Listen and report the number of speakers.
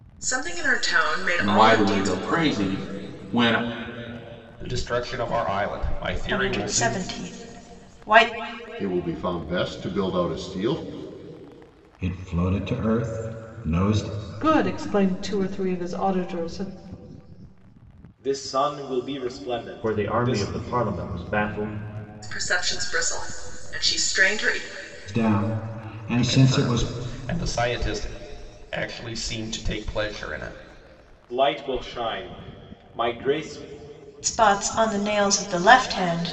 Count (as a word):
nine